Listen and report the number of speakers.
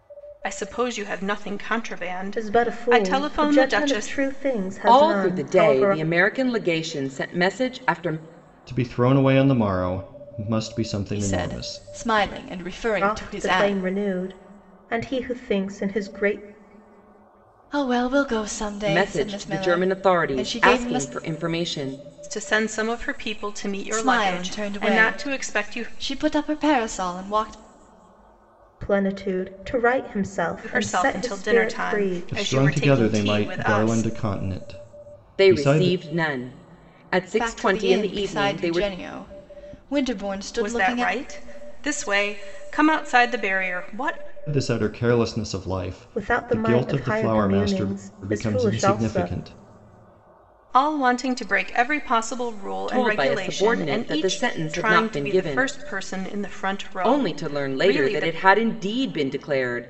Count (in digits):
5